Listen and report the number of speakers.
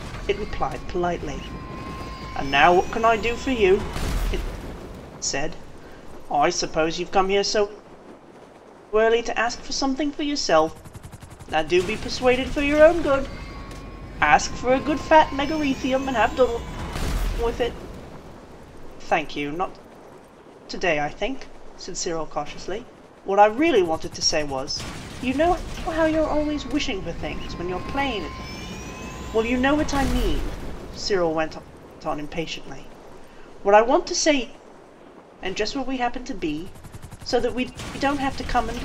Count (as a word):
one